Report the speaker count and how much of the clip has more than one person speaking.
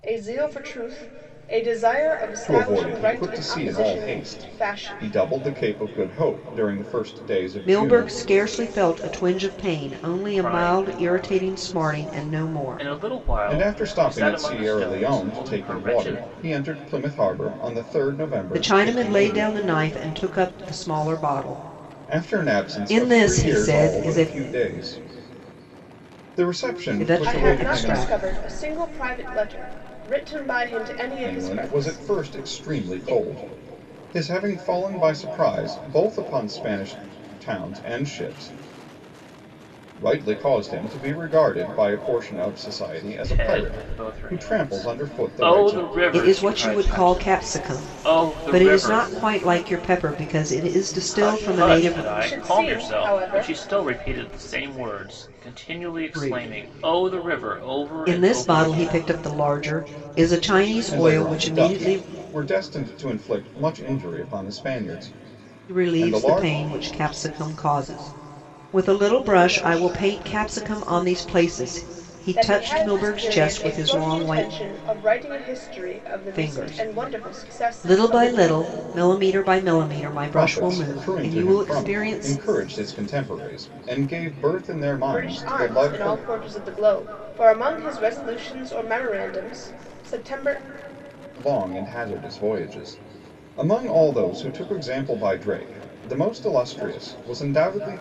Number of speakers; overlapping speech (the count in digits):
4, about 37%